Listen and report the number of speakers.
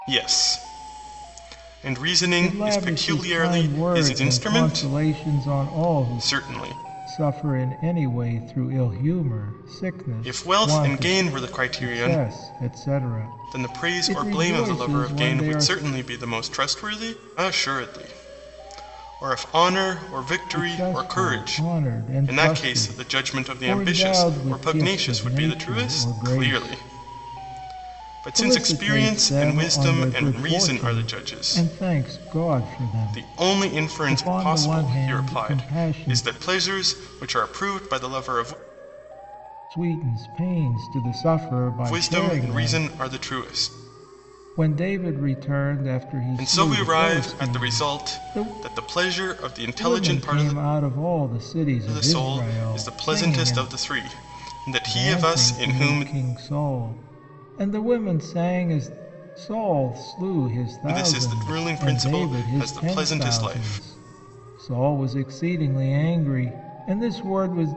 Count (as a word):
two